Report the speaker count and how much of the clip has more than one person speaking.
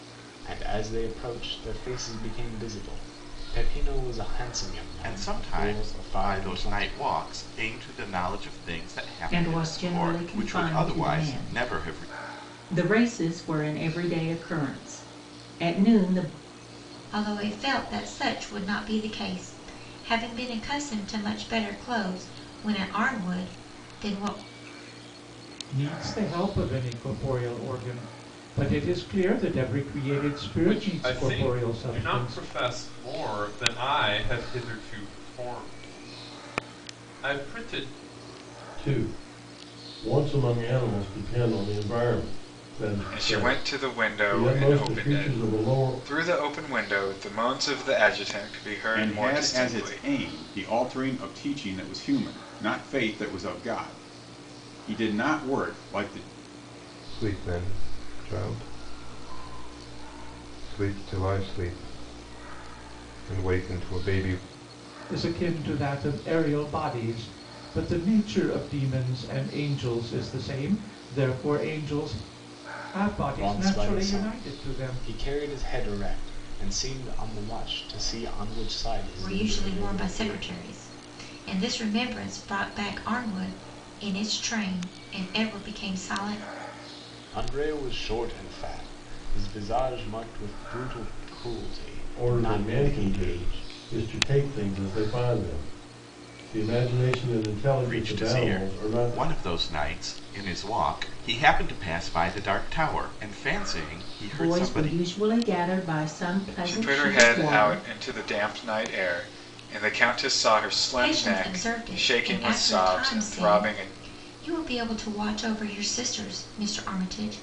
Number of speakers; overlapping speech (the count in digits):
10, about 18%